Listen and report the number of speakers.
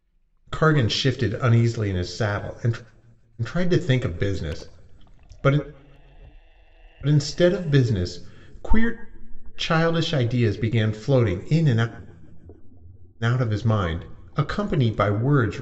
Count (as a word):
one